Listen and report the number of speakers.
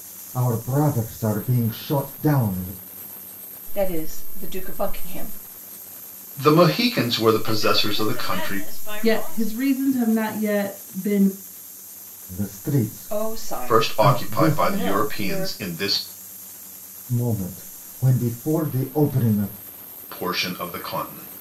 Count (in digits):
5